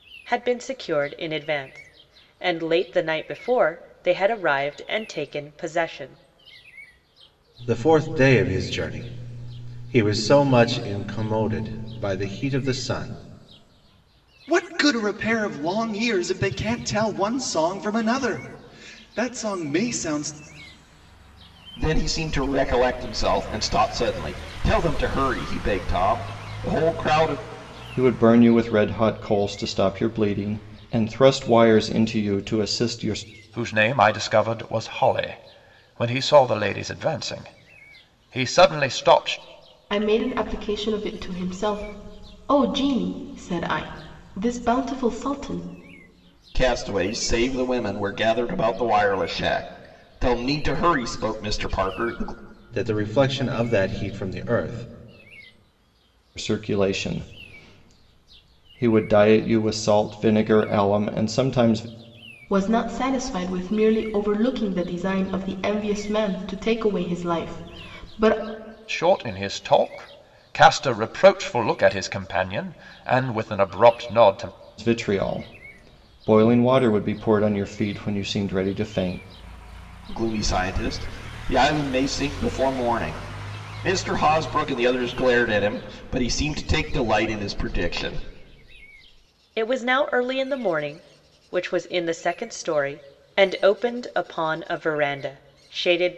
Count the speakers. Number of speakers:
7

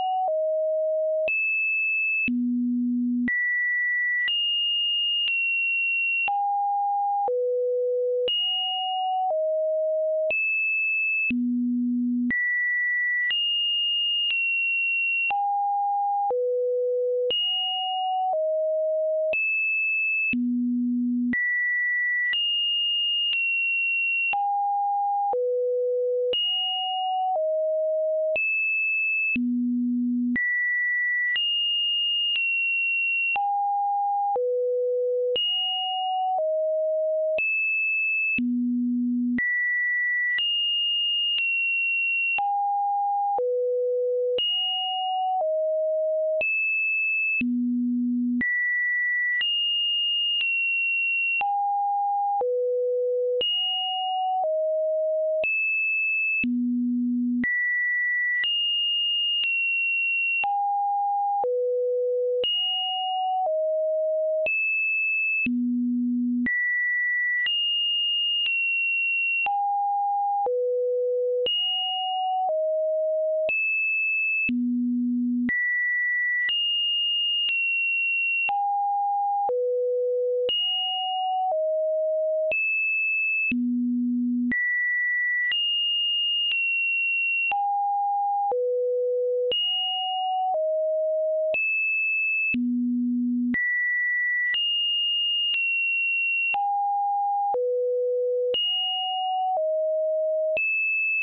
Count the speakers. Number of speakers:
0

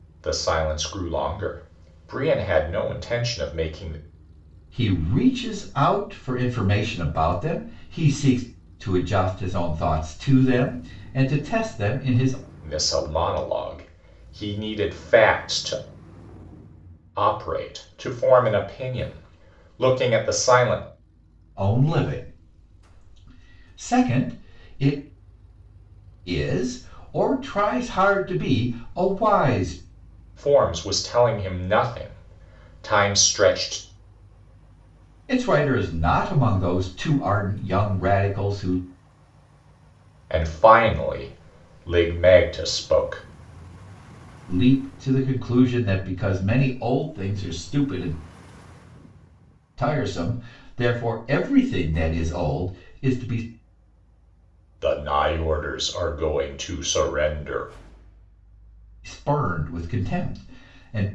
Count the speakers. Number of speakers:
2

